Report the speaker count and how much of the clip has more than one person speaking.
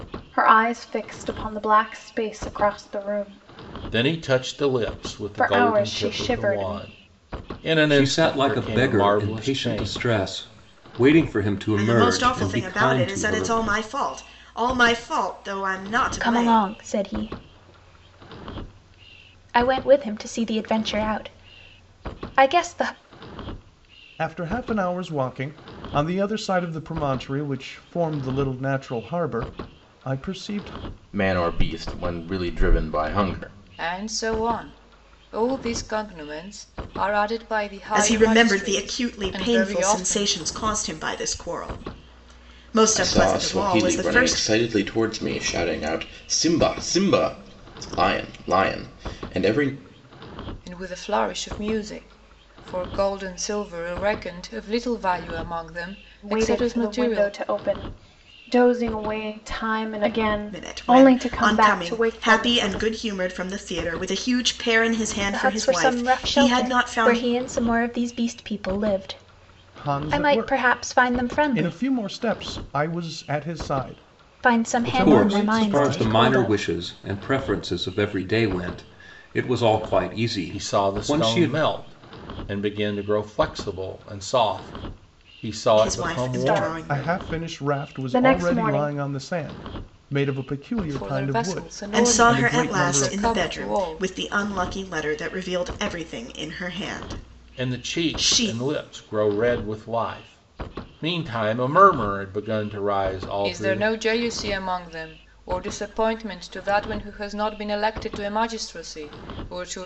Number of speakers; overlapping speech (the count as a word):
eight, about 28%